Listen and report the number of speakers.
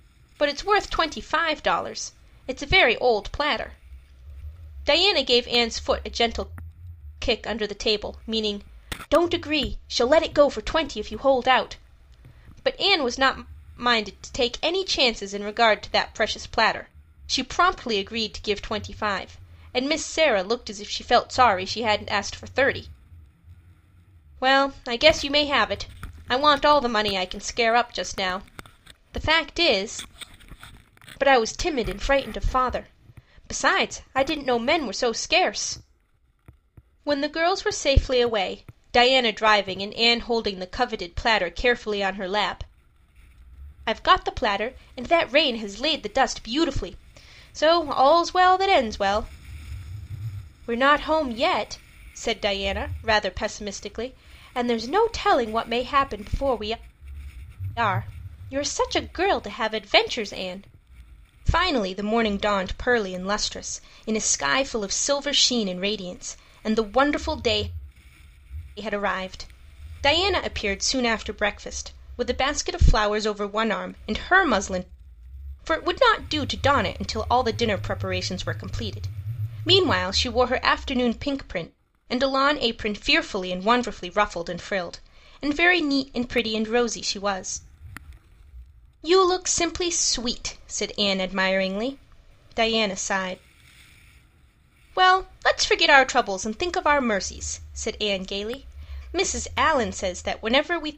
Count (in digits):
1